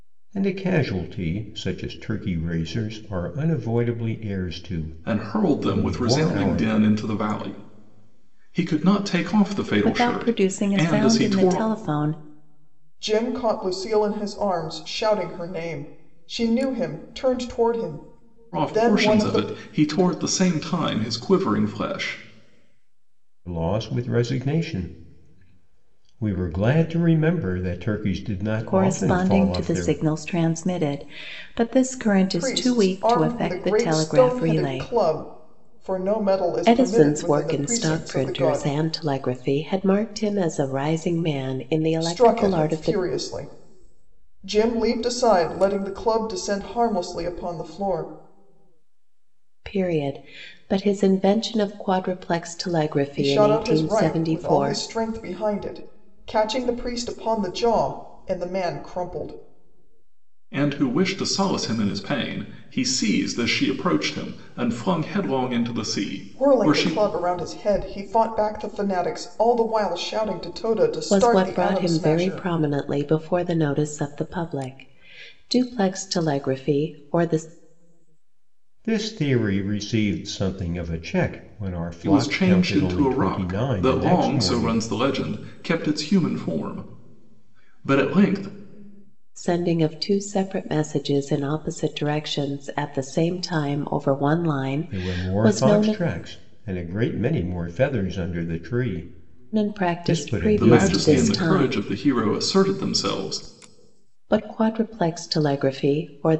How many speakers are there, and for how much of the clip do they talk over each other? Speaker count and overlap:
4, about 20%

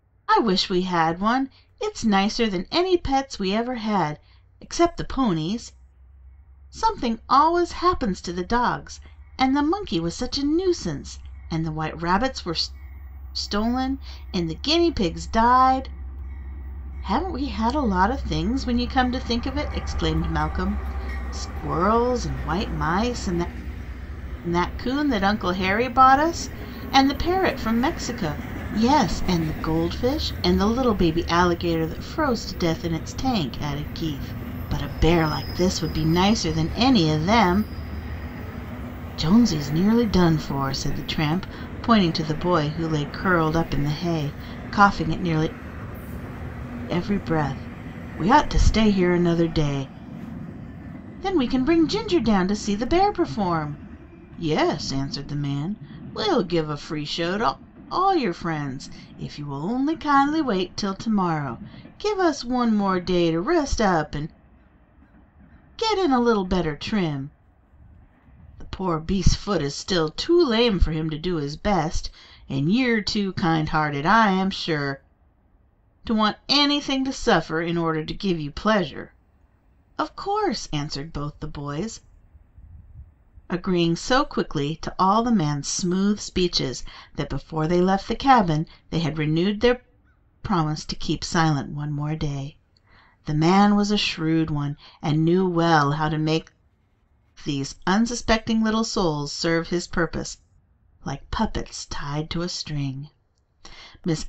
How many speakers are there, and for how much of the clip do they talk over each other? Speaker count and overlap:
1, no overlap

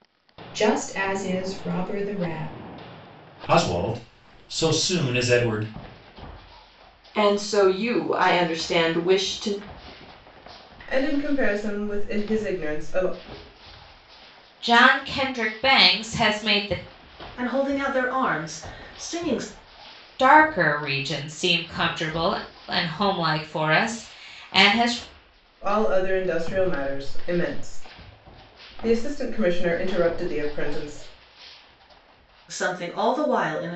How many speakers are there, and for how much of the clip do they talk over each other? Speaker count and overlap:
6, no overlap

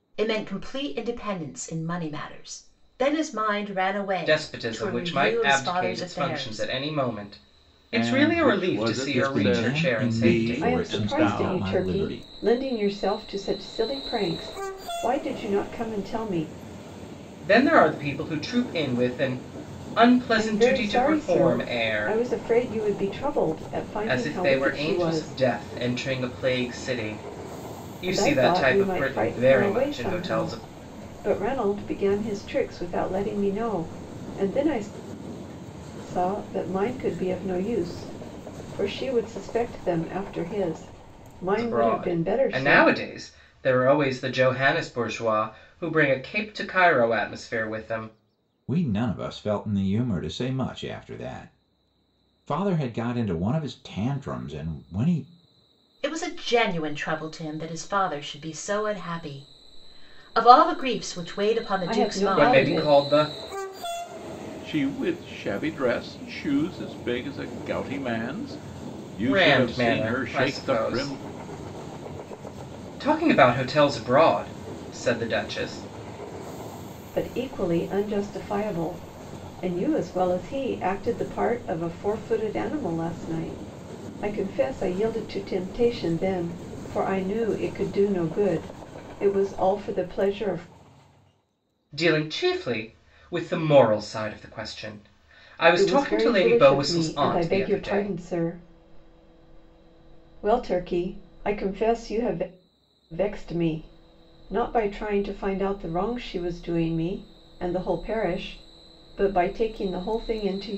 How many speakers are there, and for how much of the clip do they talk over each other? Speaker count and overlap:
5, about 18%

